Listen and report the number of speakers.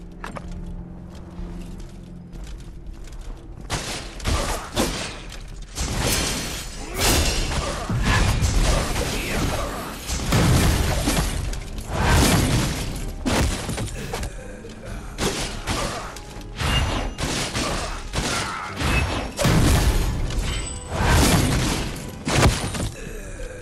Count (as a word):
zero